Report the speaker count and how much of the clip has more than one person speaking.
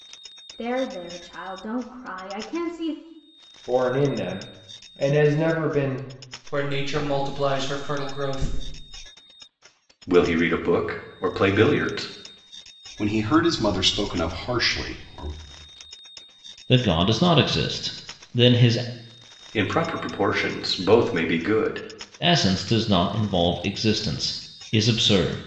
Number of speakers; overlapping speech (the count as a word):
six, no overlap